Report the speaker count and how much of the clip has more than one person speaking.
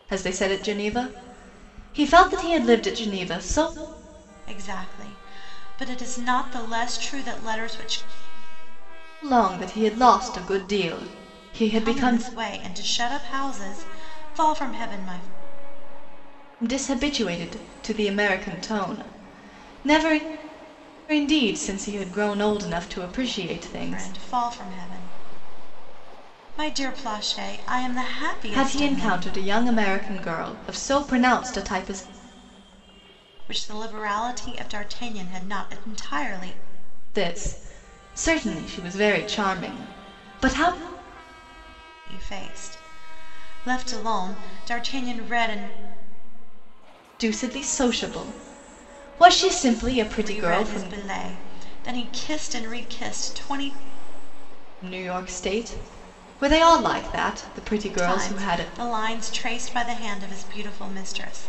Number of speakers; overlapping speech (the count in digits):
2, about 5%